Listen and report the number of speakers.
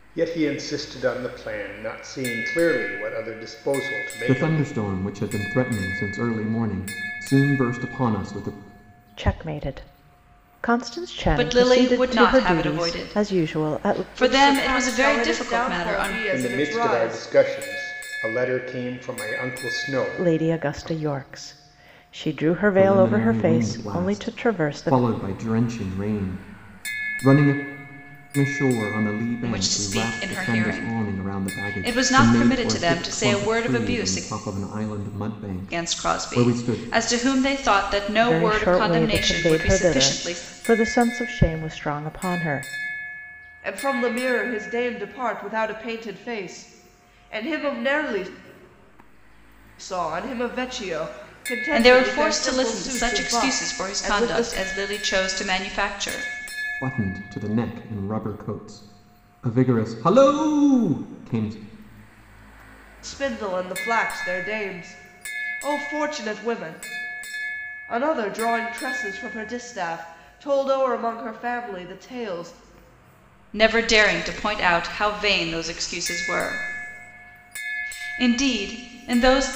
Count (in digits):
5